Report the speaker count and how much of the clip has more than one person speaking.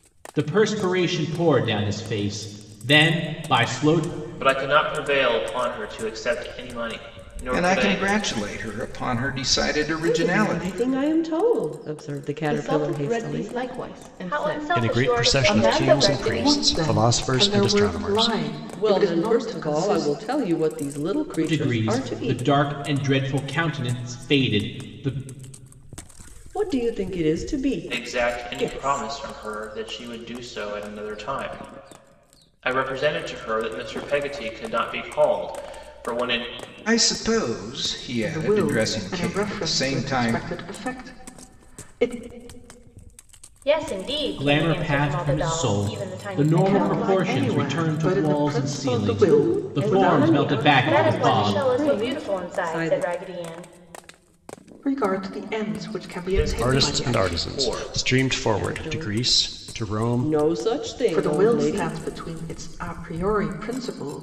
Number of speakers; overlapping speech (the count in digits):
8, about 40%